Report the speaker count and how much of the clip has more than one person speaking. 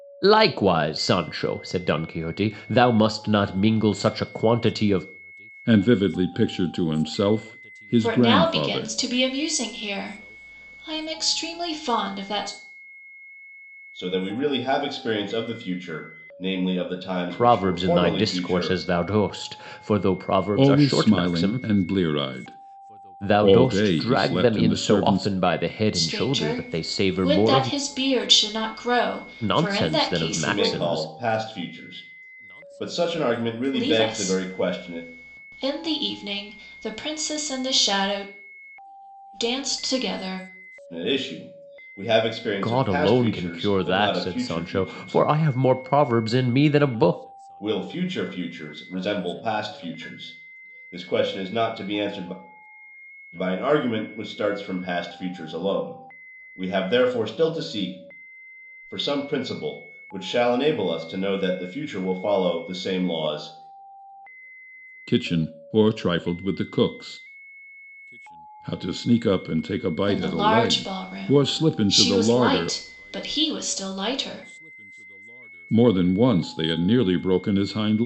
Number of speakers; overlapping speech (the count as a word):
four, about 21%